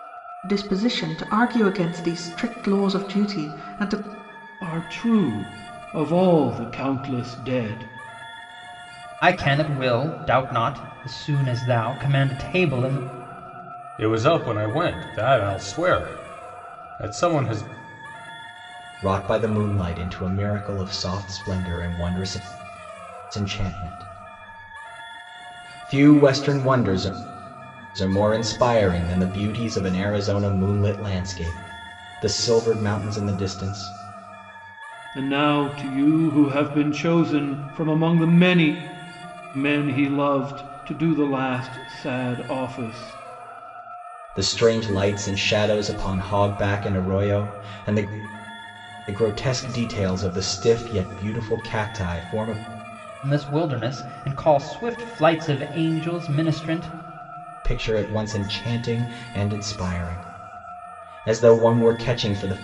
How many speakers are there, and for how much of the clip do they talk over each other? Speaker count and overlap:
five, no overlap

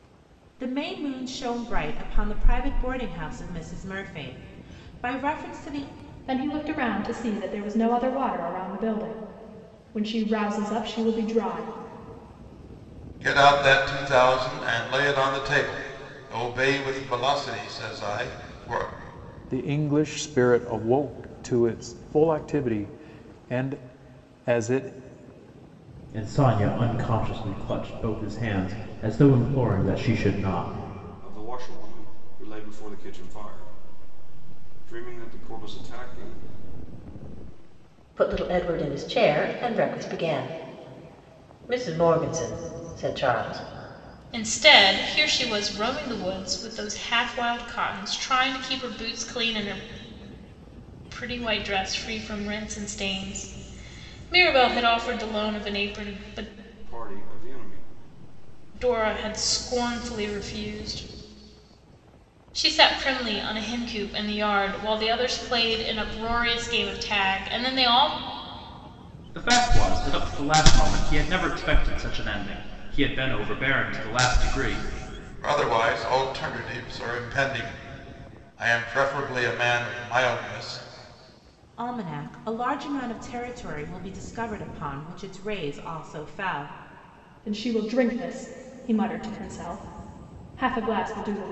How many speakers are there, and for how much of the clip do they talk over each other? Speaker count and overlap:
eight, no overlap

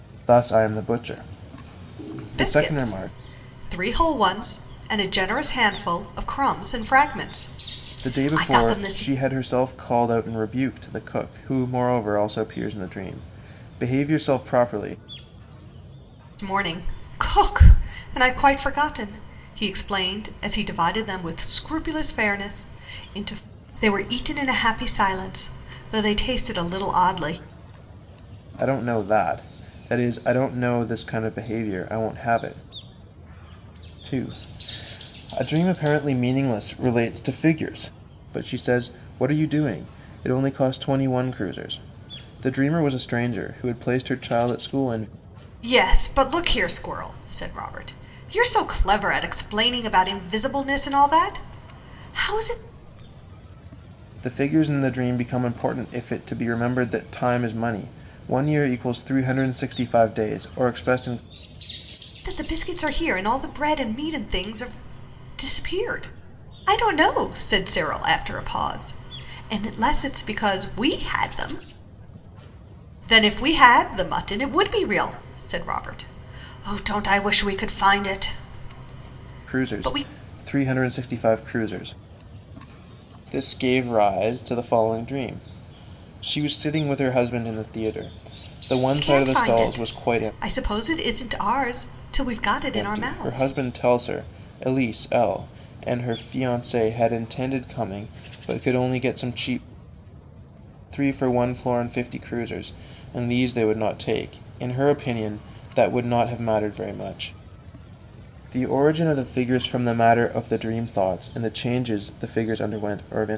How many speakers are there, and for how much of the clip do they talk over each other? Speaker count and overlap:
two, about 4%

